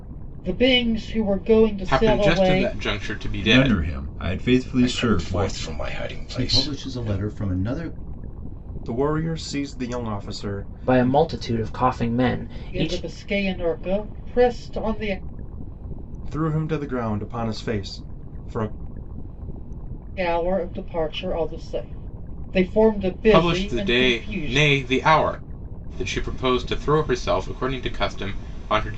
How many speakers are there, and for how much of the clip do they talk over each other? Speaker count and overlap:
7, about 18%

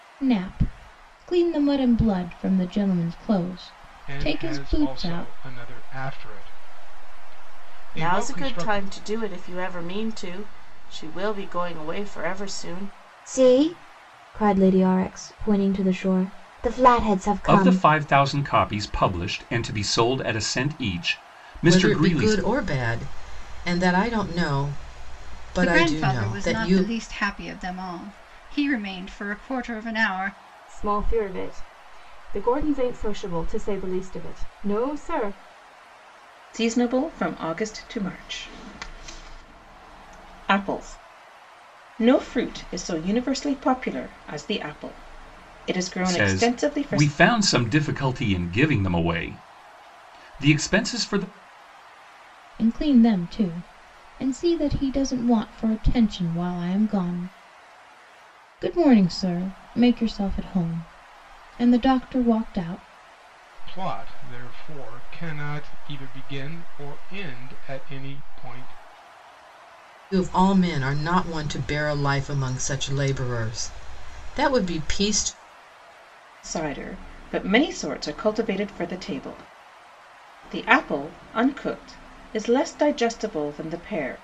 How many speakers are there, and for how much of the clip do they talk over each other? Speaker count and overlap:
9, about 7%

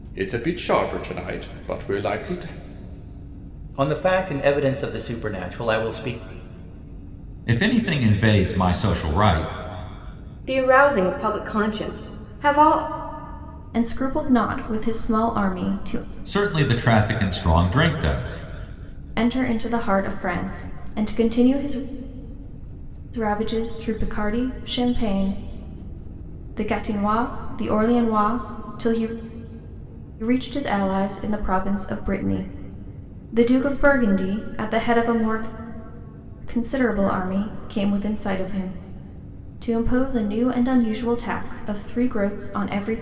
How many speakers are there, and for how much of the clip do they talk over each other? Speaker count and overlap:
5, no overlap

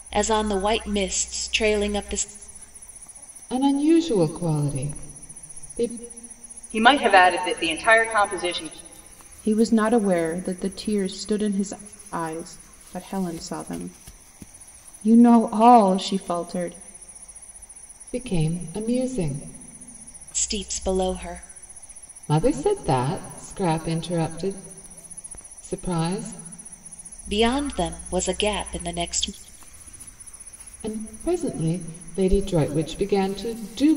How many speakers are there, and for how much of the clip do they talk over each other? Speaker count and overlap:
4, no overlap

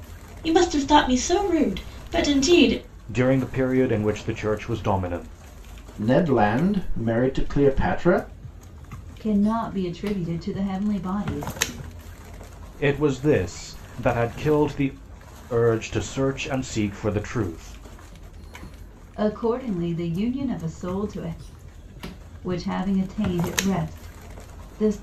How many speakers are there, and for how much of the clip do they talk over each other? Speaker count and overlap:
4, no overlap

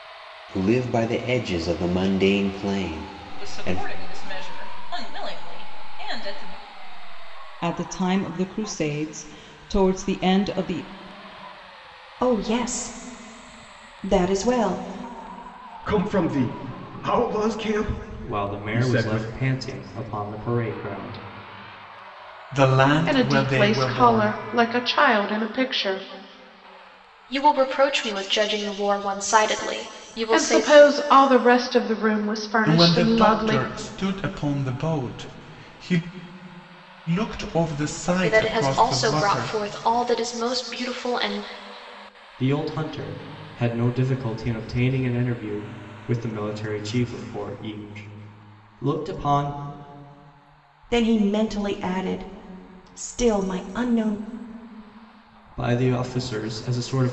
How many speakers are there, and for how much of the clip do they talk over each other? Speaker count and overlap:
9, about 10%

